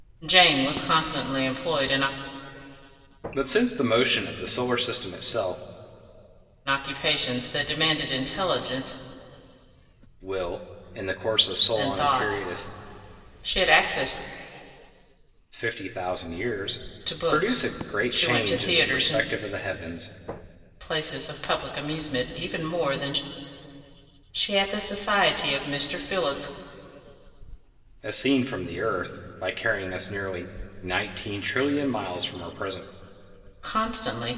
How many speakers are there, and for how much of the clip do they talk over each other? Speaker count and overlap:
2, about 9%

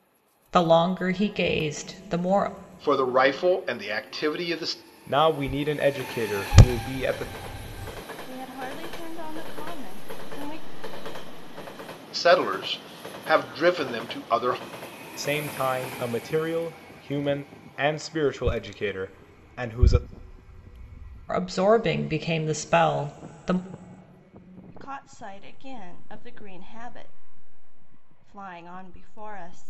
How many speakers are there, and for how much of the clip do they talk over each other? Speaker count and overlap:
4, no overlap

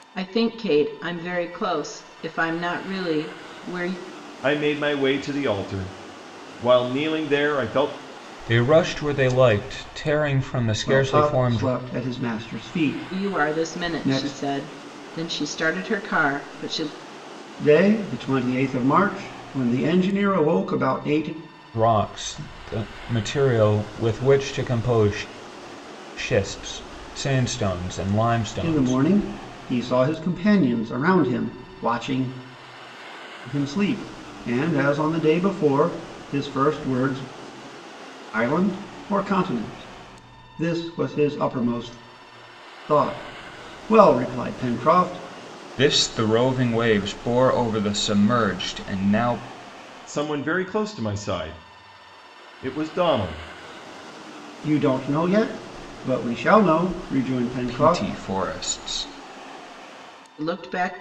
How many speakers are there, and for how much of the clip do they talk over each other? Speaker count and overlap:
4, about 5%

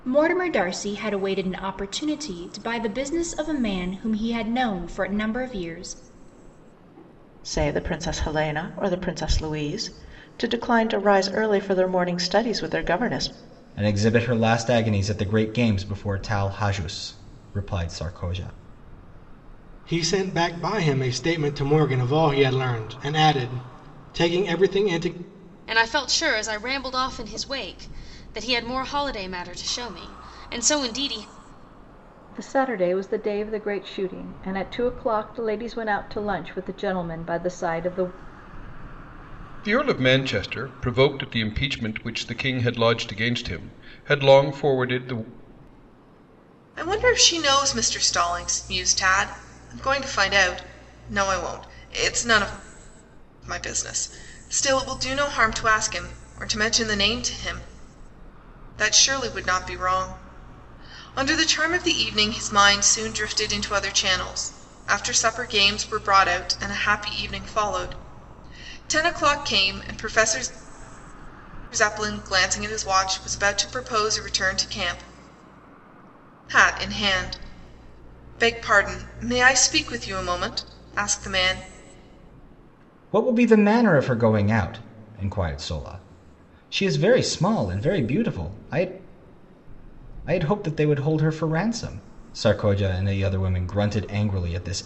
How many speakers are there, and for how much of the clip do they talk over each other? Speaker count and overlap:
8, no overlap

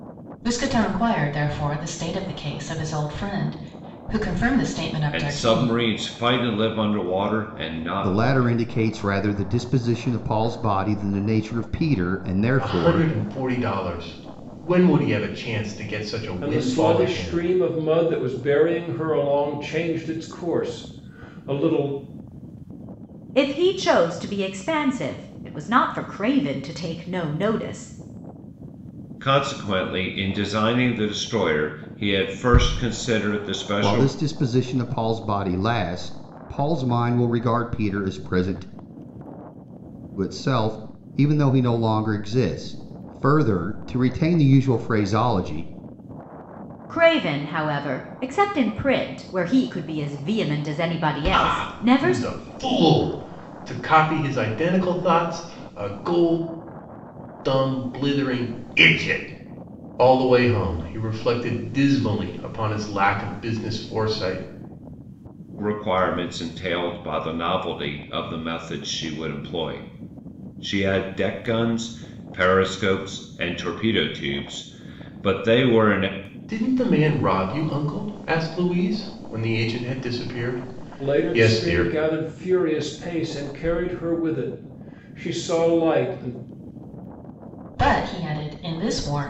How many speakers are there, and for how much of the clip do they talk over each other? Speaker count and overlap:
6, about 6%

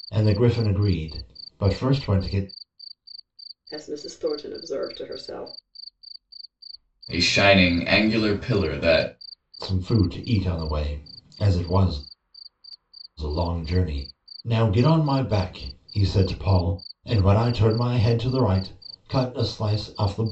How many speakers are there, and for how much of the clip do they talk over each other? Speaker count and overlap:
3, no overlap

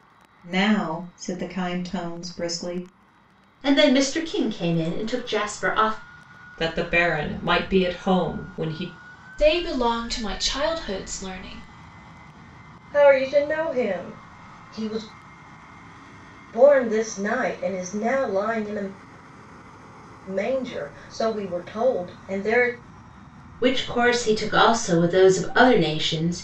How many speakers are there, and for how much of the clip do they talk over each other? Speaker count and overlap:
5, no overlap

